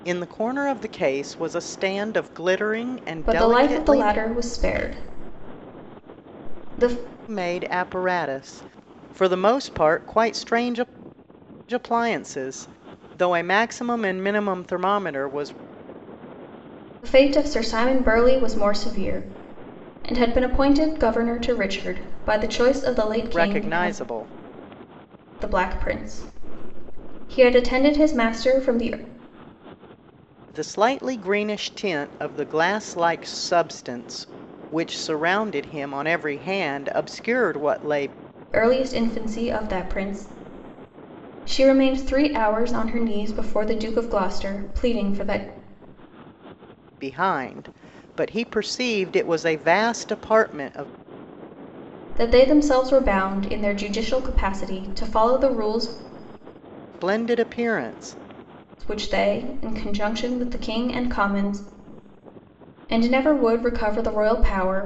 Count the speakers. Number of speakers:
2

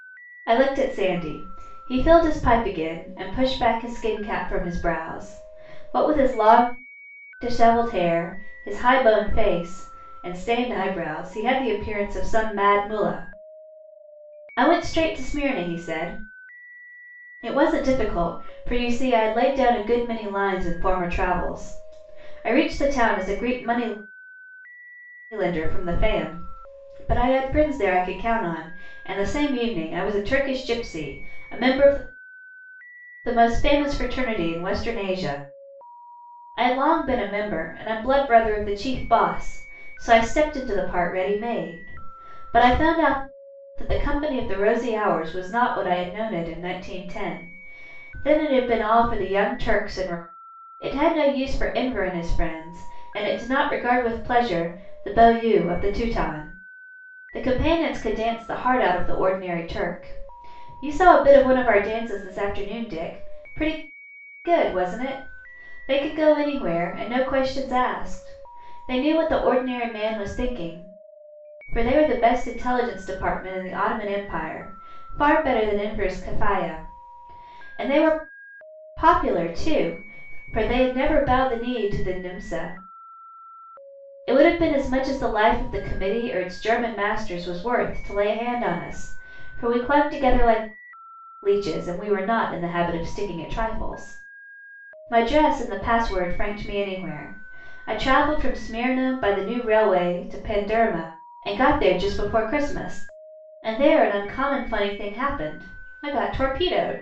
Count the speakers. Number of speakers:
1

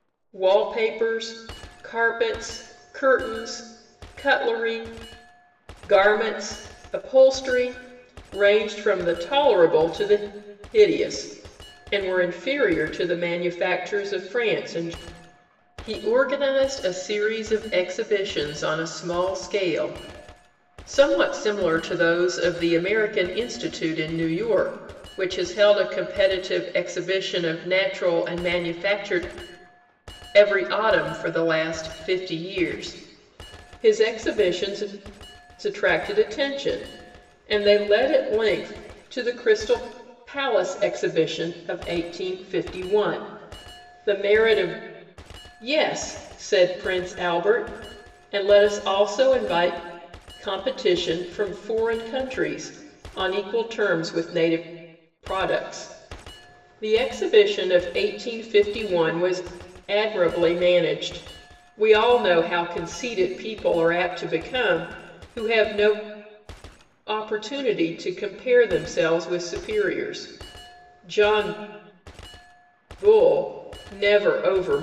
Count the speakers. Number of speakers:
1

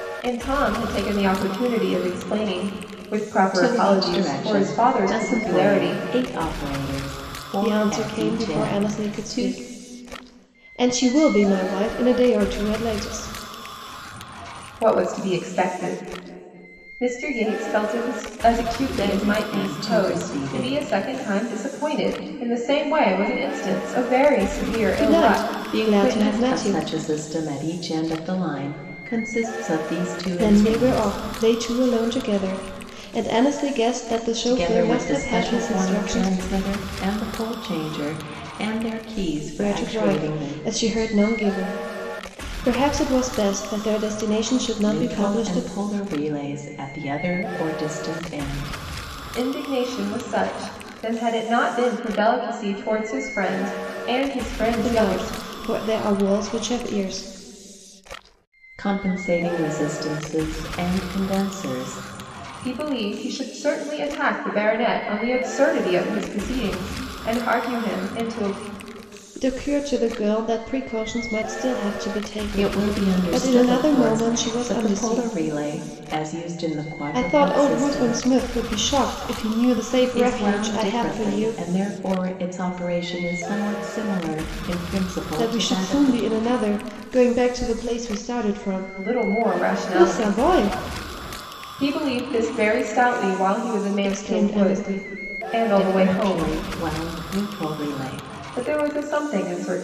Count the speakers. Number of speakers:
3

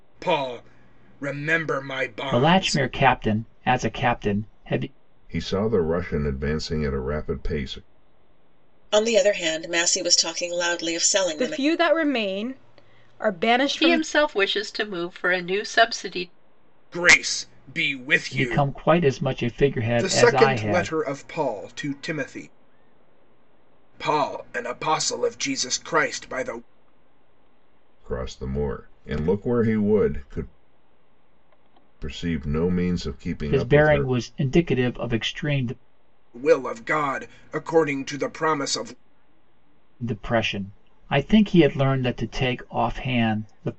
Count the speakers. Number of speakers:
6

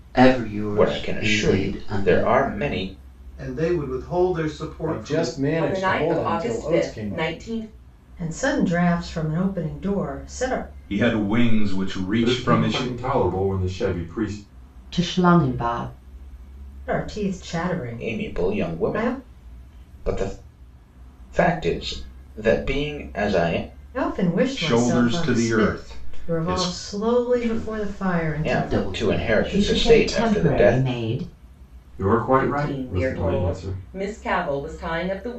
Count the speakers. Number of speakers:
9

